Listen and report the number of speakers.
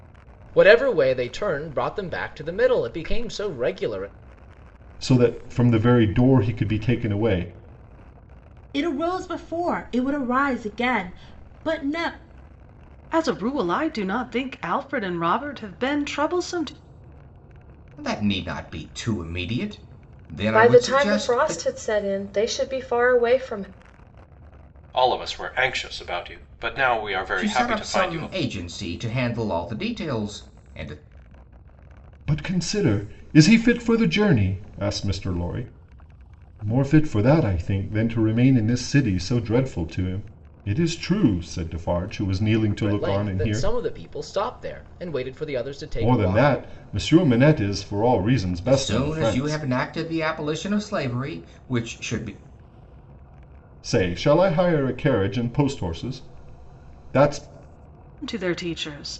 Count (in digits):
7